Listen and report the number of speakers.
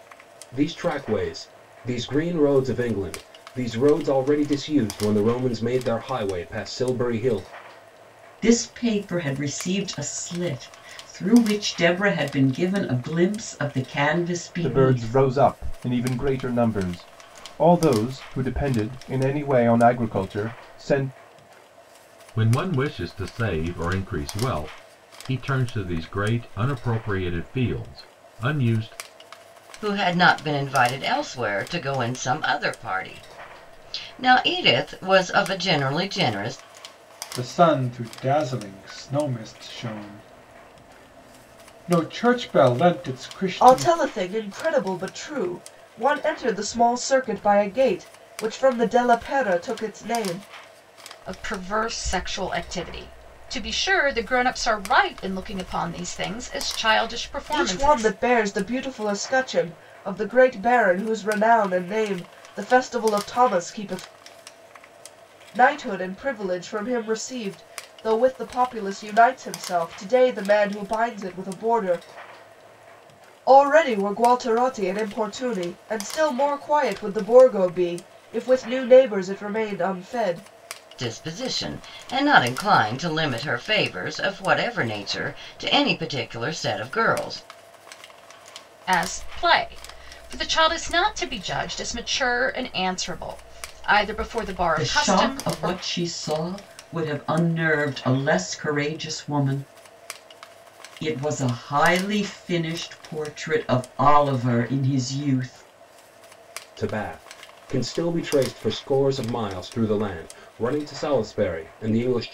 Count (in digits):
8